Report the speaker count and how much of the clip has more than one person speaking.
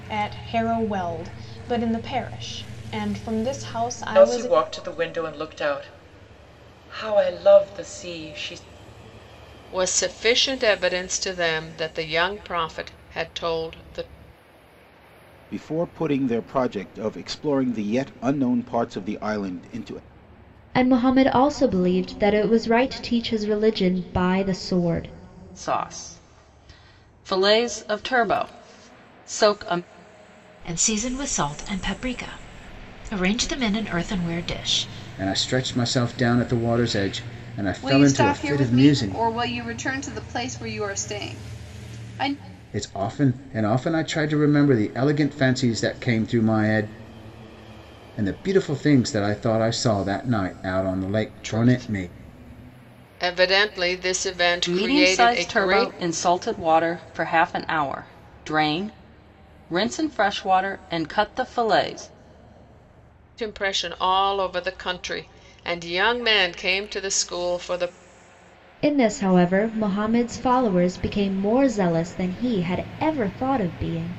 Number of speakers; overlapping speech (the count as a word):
nine, about 5%